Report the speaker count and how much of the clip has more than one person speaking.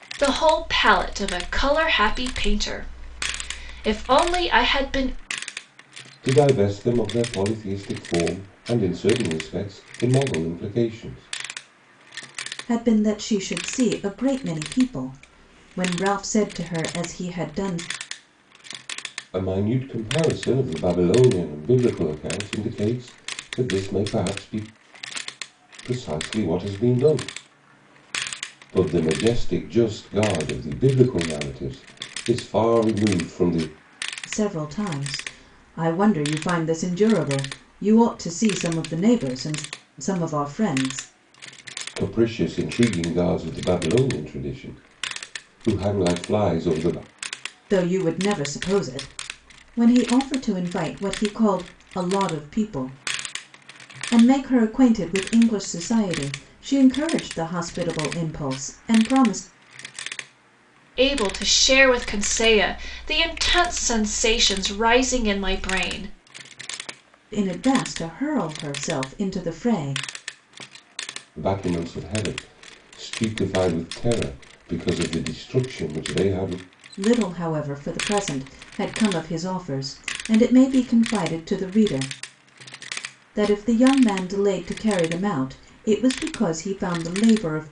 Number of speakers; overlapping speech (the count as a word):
three, no overlap